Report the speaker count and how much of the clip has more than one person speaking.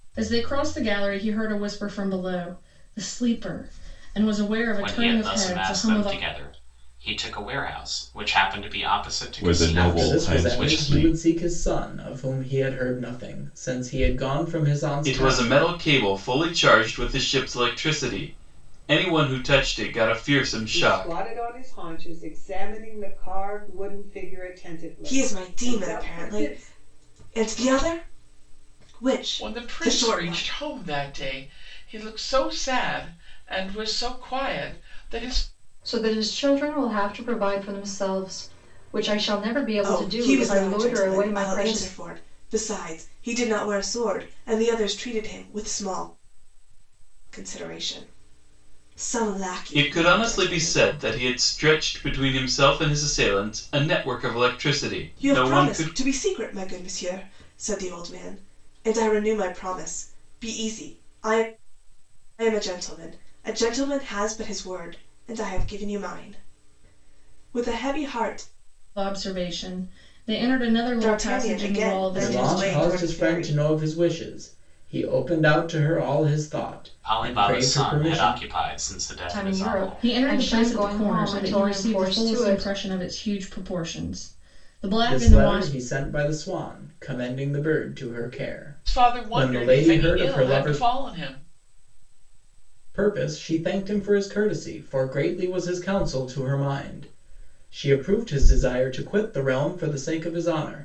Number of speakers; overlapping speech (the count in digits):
9, about 22%